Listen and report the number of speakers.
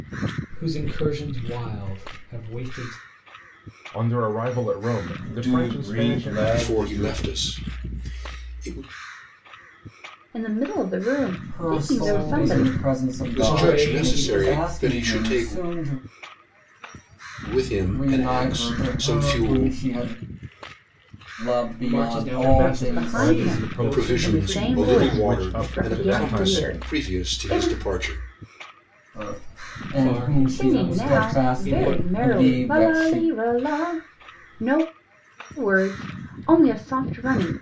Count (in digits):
6